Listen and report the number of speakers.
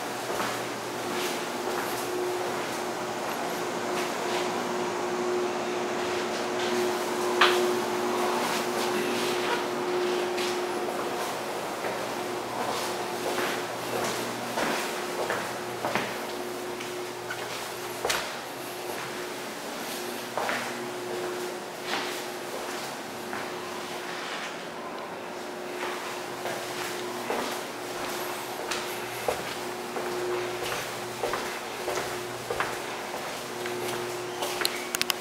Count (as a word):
zero